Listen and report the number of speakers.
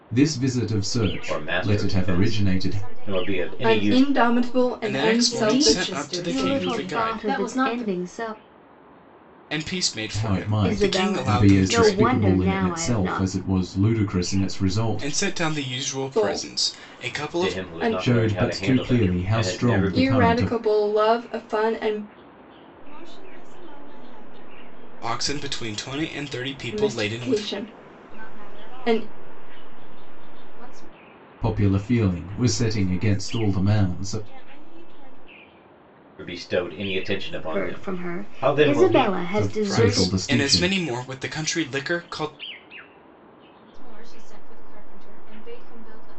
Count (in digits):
8